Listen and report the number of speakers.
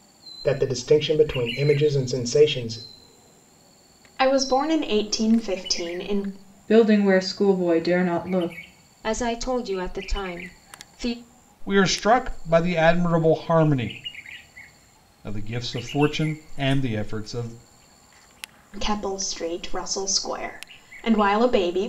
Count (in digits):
5